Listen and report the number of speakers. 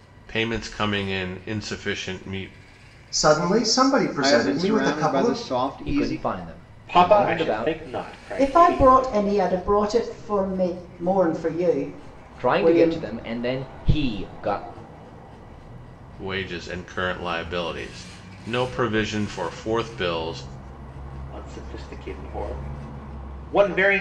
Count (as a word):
six